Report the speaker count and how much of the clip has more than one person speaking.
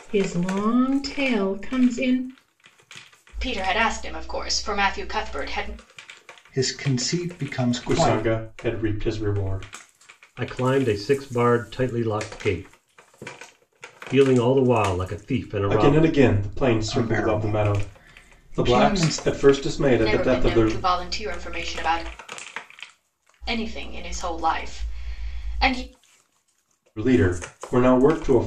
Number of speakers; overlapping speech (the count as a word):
five, about 12%